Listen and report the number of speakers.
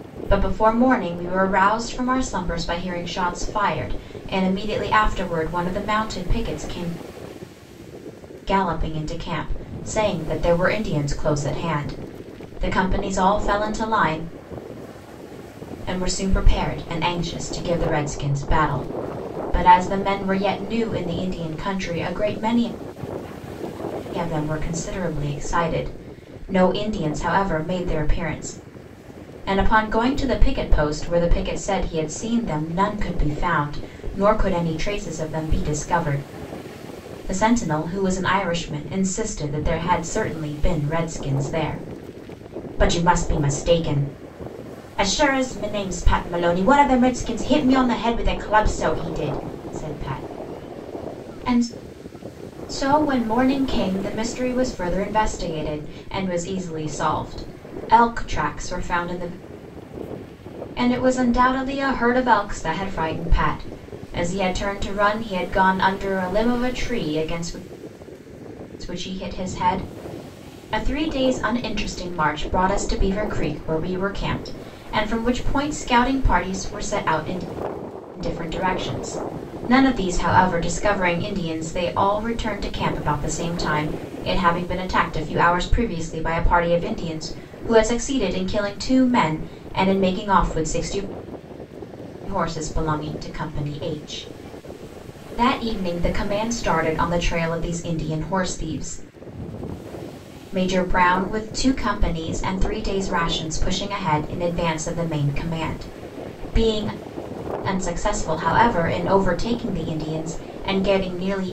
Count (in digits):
1